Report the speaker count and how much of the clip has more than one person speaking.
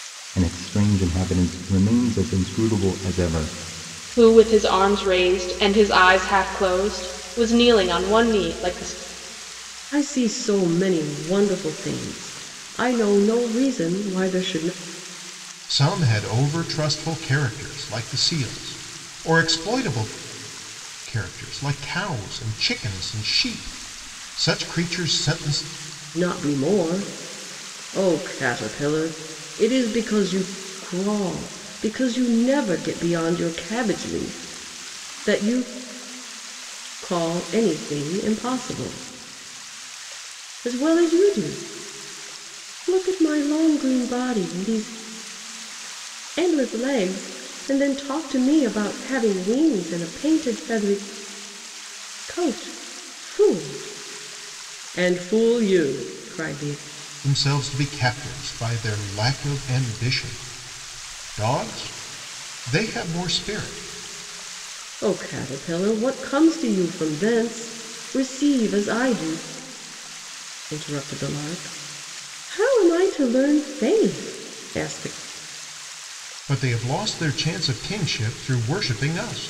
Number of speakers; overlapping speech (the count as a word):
four, no overlap